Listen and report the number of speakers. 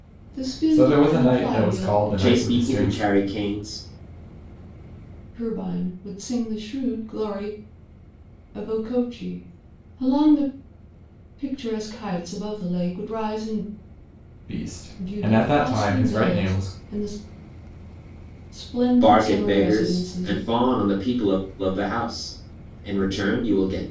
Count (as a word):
three